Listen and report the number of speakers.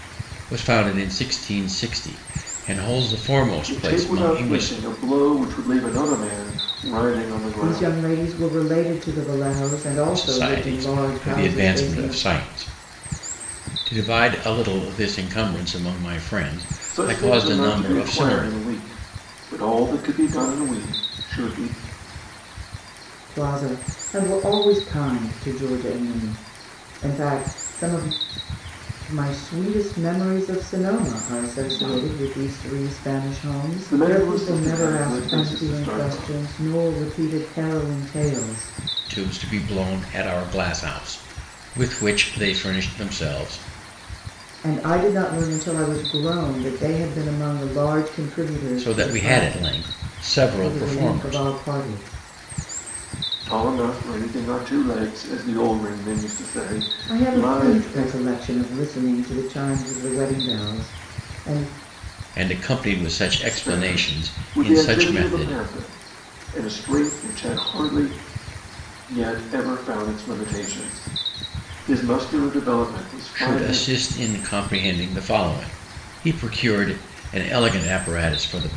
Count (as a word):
three